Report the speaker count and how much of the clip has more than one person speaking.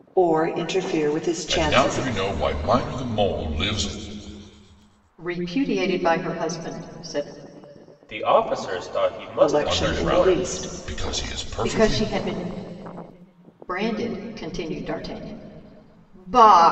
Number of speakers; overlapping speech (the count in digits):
4, about 20%